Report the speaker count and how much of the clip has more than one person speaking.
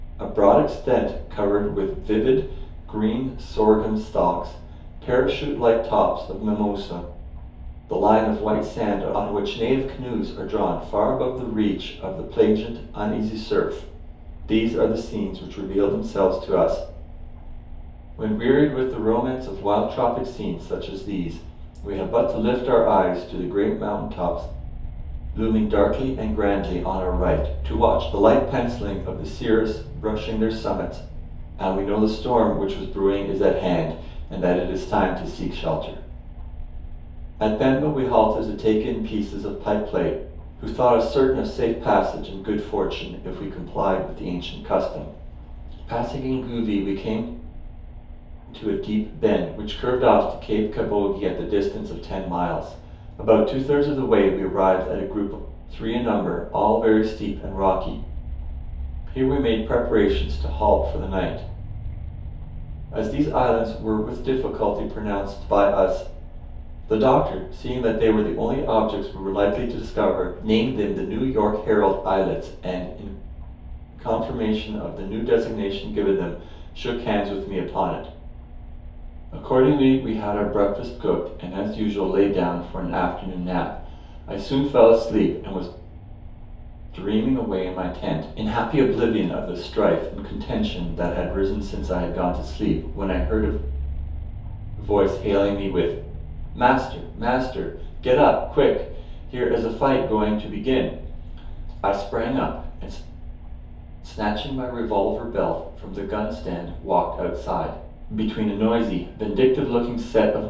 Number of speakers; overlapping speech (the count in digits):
1, no overlap